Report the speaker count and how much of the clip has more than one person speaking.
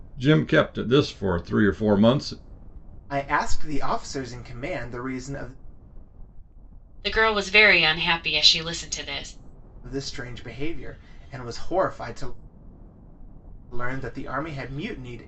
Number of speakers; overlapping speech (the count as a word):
three, no overlap